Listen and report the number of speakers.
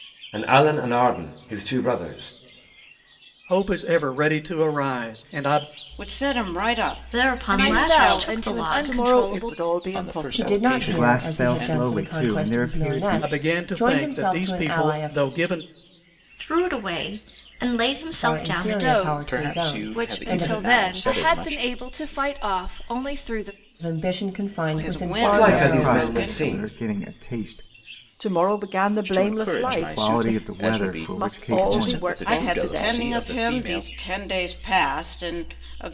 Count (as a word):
nine